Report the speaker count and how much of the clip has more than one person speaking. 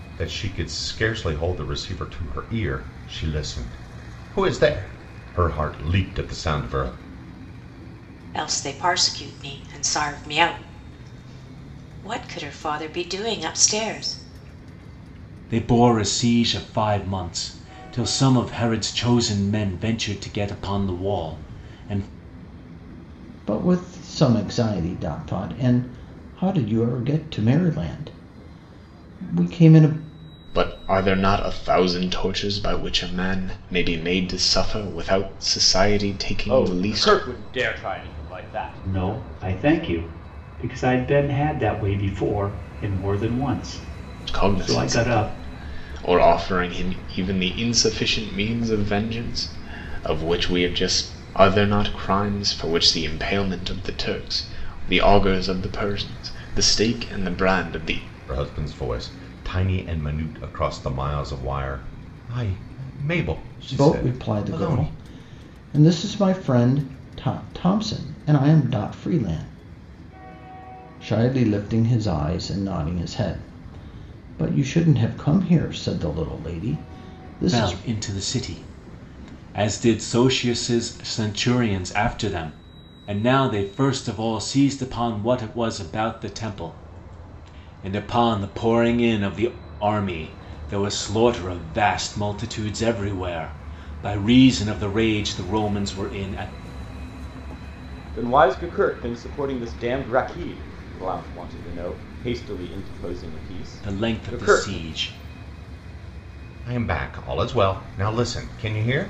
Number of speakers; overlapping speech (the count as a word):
seven, about 5%